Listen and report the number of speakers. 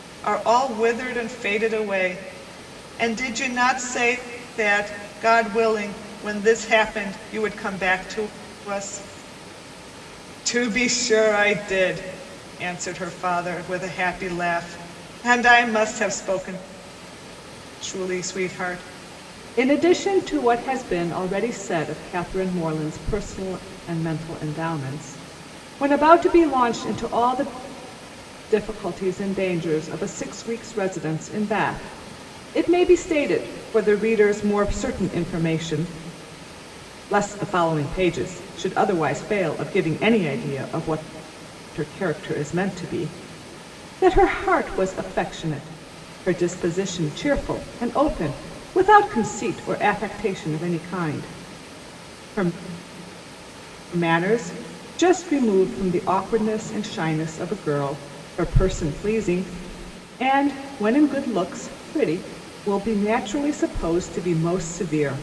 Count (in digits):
1